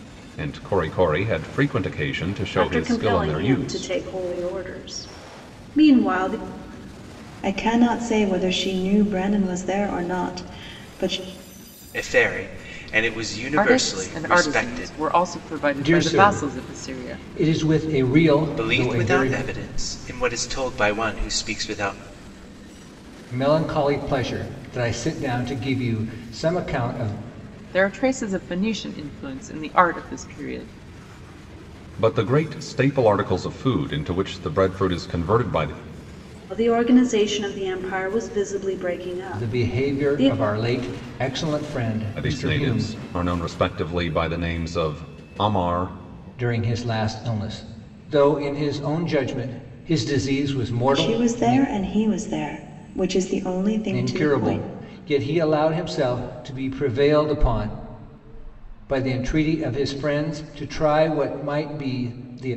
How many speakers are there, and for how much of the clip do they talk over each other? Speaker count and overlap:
6, about 14%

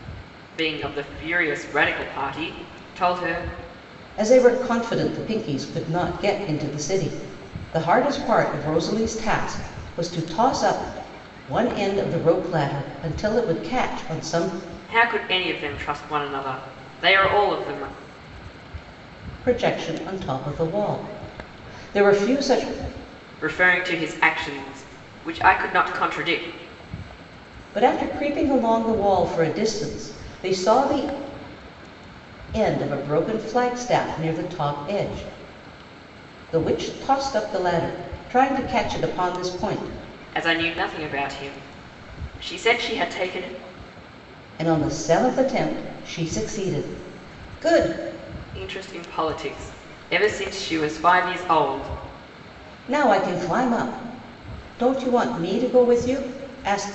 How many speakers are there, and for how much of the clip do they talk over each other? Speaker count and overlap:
2, no overlap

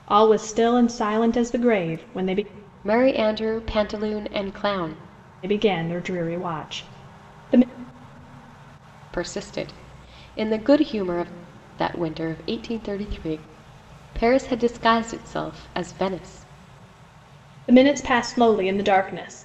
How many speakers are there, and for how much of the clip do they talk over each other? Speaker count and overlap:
2, no overlap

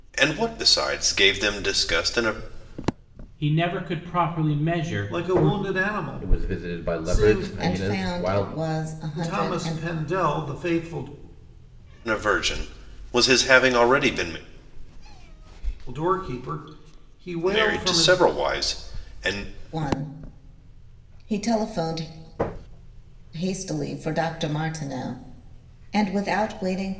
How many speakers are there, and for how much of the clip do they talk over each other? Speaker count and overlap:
5, about 16%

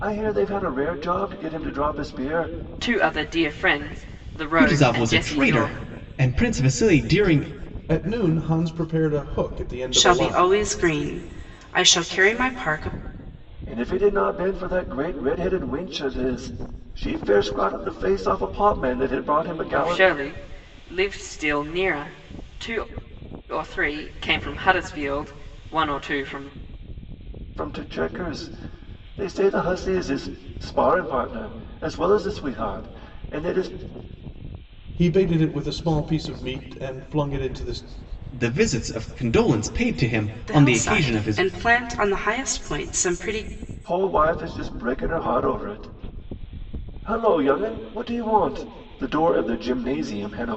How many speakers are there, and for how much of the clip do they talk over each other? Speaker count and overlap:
5, about 7%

